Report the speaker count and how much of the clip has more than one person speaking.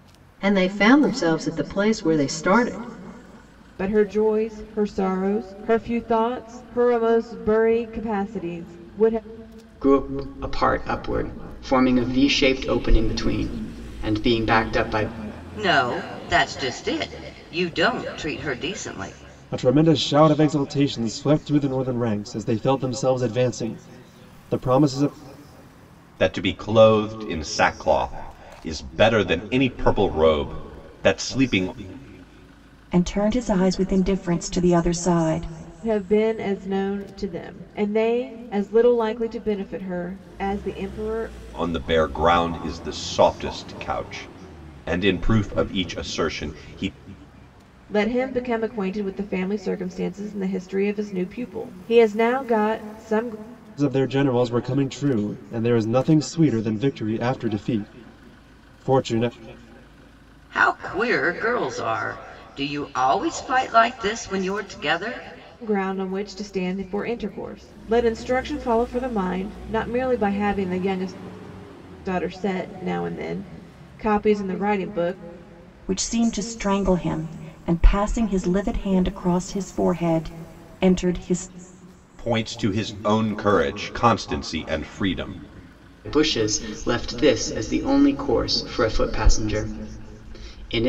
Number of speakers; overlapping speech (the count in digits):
7, no overlap